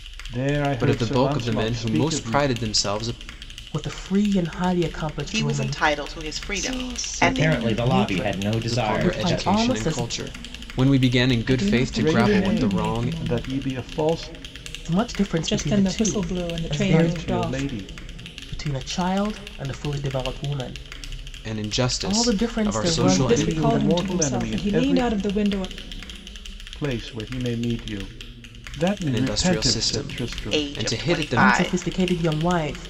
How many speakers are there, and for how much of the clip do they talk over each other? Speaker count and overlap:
six, about 49%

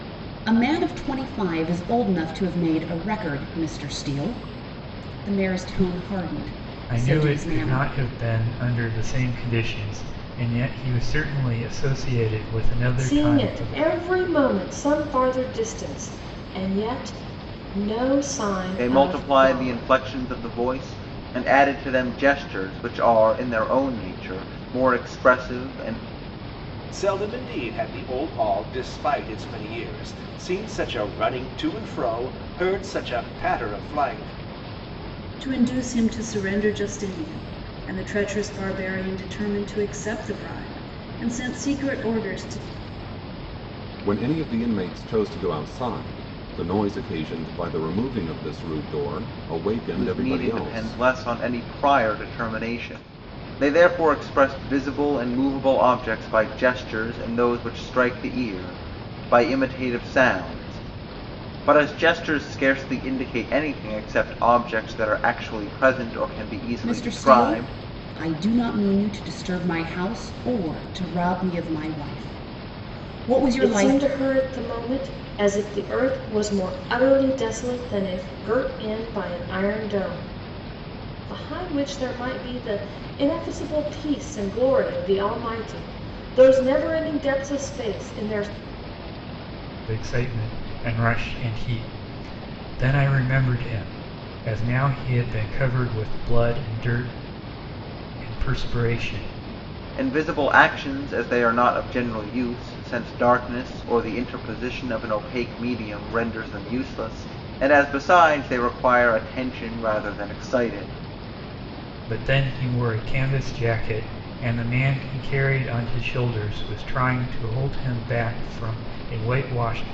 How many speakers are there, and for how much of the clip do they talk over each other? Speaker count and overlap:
seven, about 5%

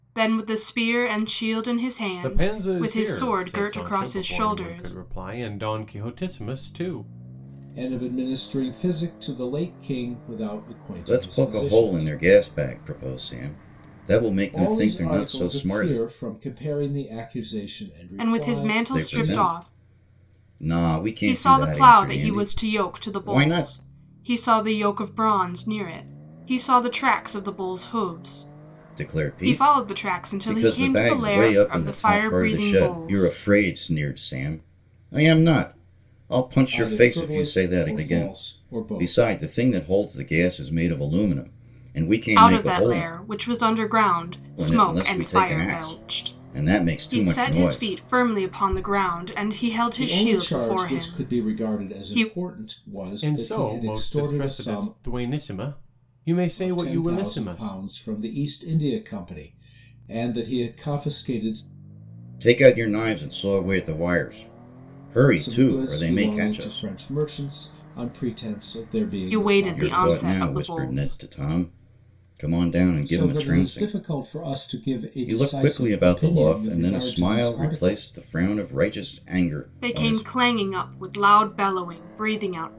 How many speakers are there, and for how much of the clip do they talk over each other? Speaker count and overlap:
four, about 41%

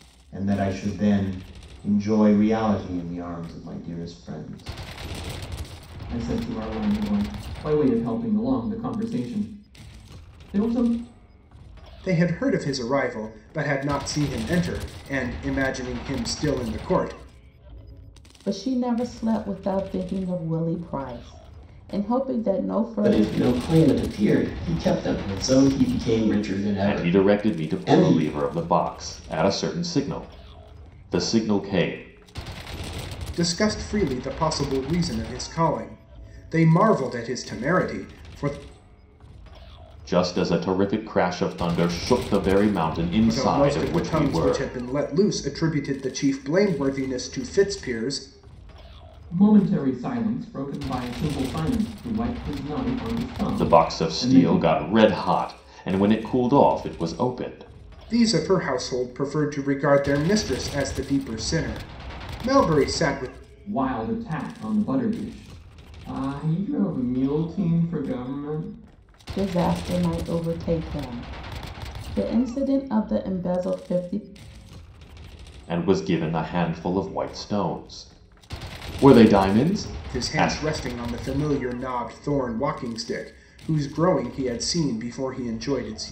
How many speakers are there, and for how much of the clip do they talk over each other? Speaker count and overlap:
six, about 6%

